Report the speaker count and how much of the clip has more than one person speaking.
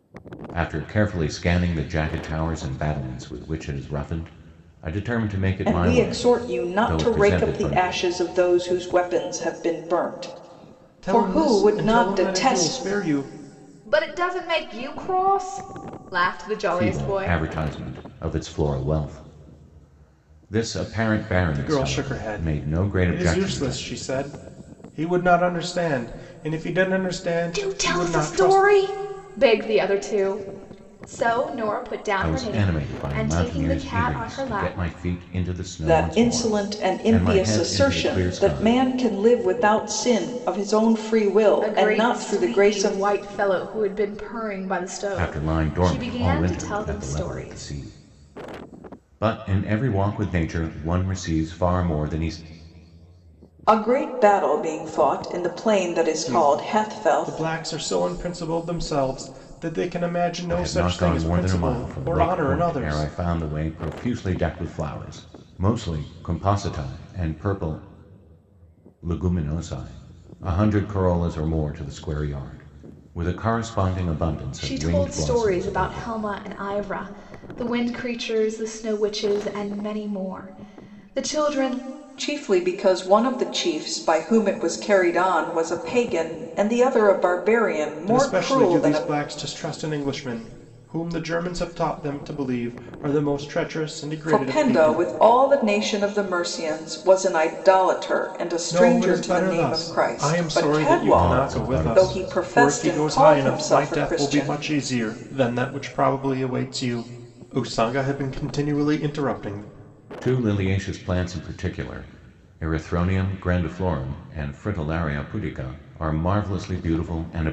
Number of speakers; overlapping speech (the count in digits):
4, about 27%